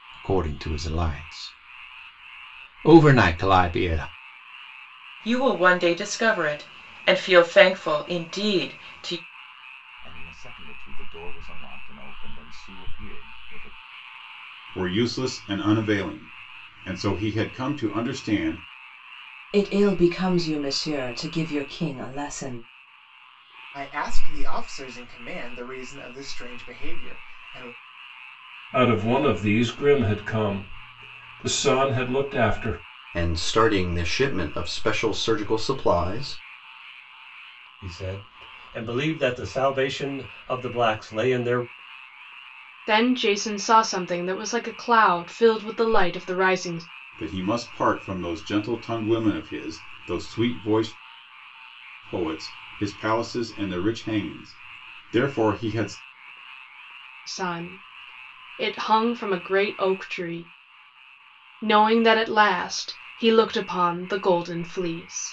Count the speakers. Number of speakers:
10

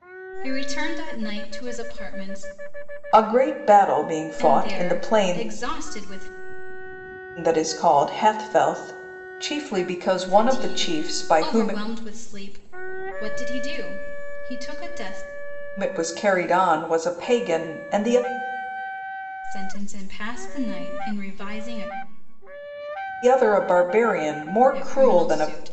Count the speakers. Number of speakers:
2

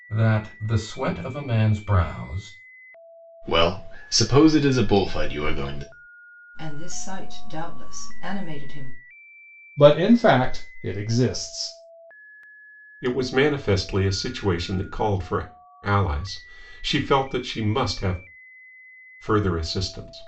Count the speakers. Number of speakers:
5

